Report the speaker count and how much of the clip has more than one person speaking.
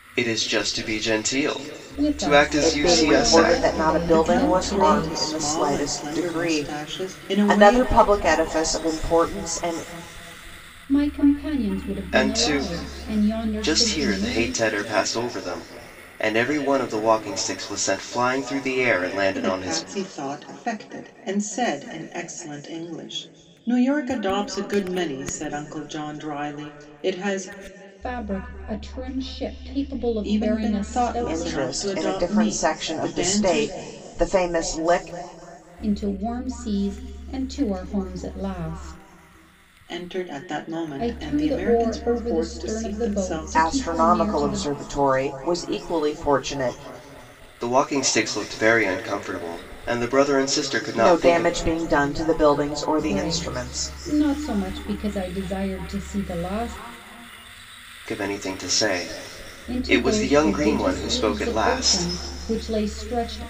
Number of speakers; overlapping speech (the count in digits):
4, about 32%